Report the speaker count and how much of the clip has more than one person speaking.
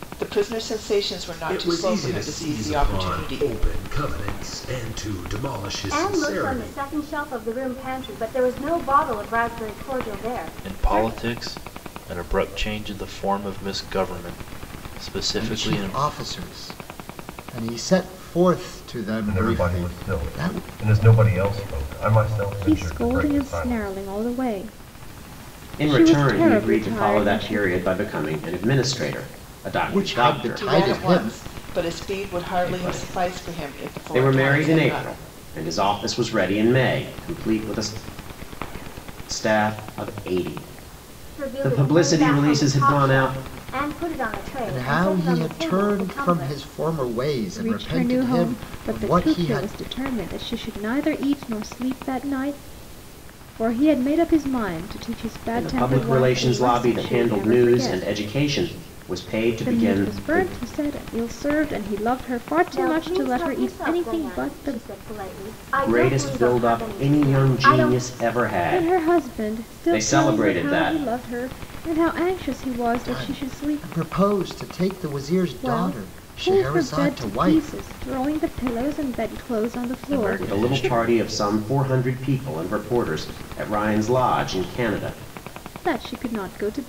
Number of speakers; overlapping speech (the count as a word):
eight, about 39%